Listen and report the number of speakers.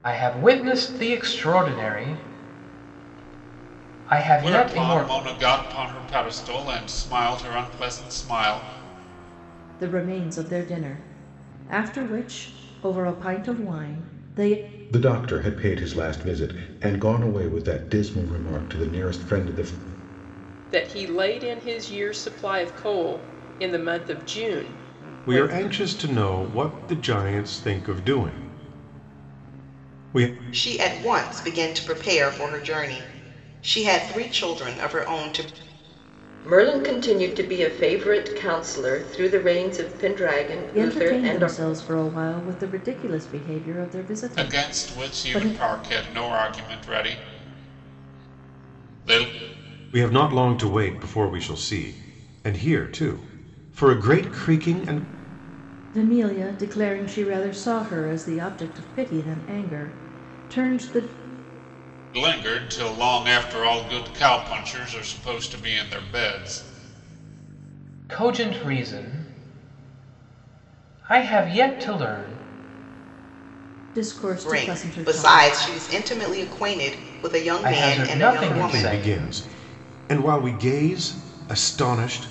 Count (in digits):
8